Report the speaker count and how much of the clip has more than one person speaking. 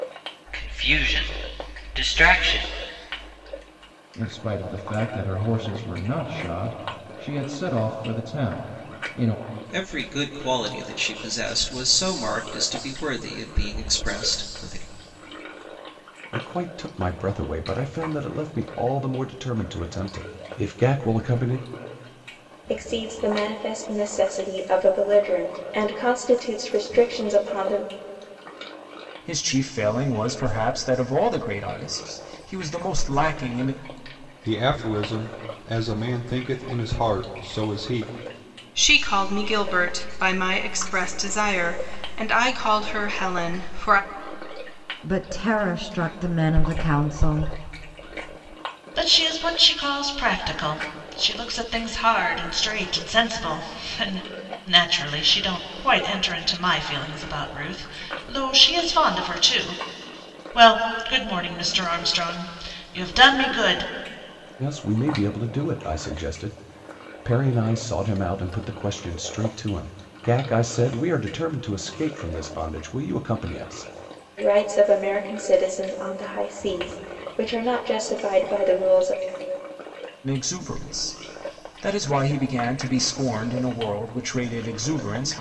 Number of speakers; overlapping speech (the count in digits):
10, no overlap